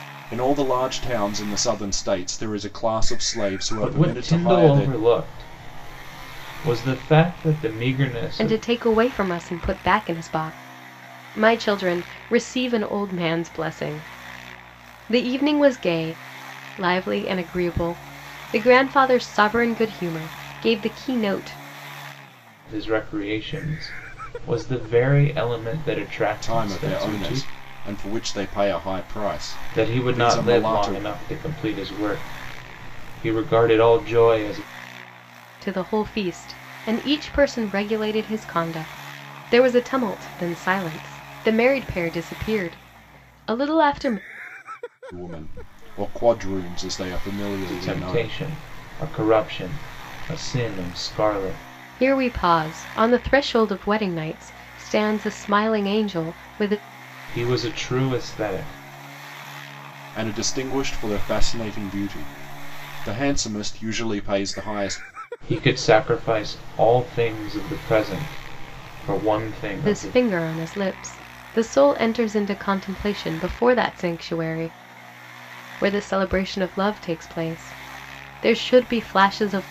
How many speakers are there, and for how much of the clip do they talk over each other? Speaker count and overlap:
3, about 6%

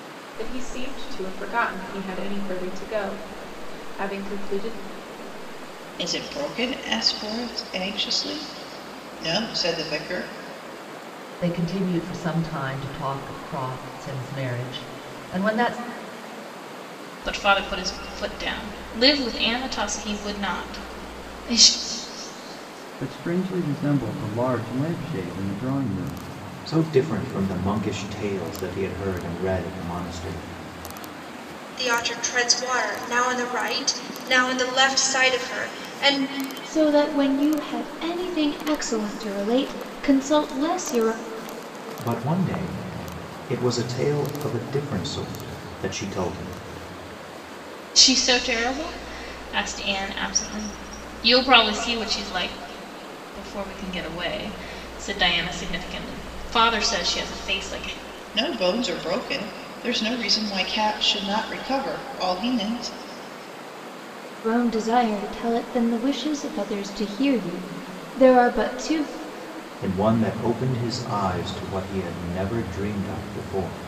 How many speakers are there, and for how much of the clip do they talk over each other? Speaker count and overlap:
8, no overlap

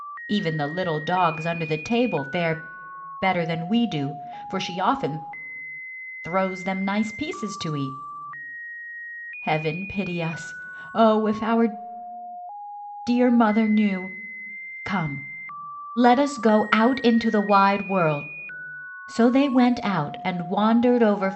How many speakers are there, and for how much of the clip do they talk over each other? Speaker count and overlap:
1, no overlap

